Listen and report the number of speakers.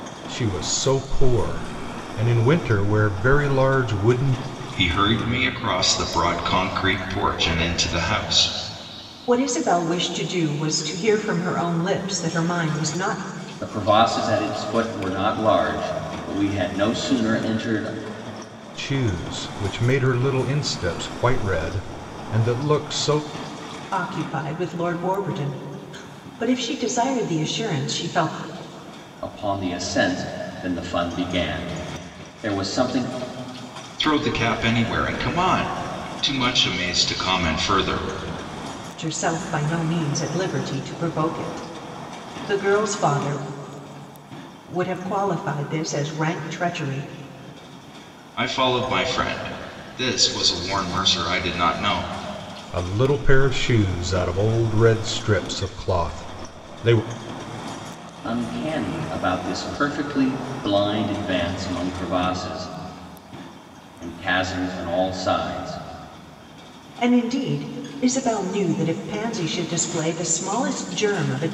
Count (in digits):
4